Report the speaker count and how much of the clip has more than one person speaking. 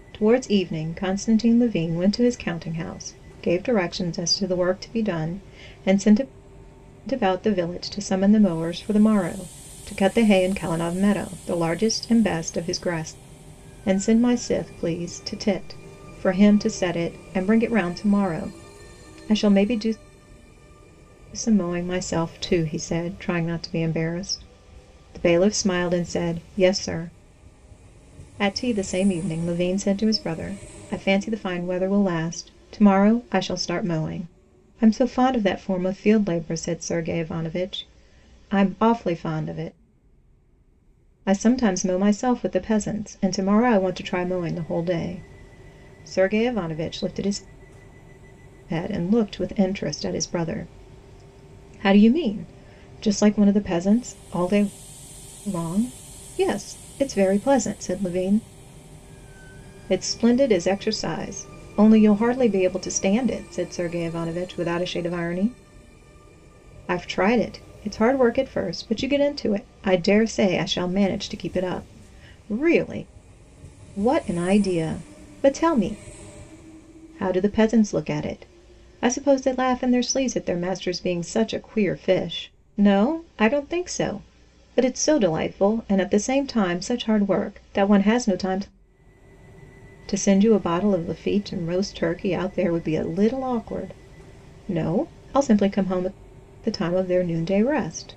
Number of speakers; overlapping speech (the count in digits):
1, no overlap